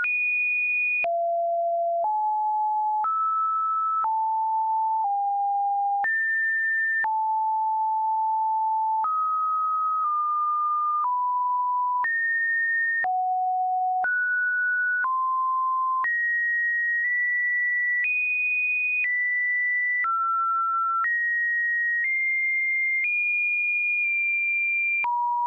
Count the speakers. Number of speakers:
zero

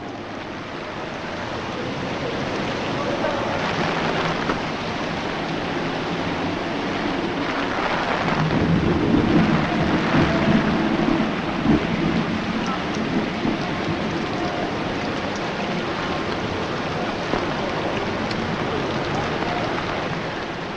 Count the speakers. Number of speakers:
zero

